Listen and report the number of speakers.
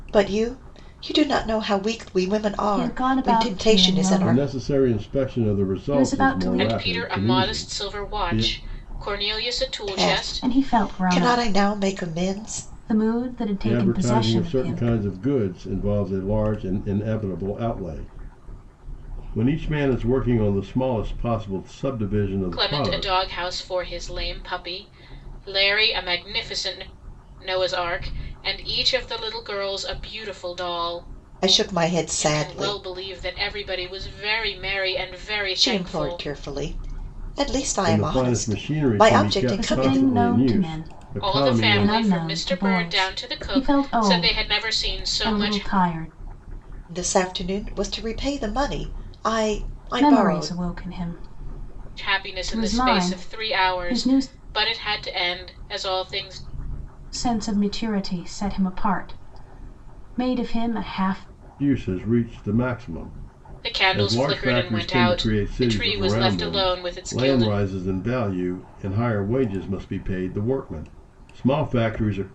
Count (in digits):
4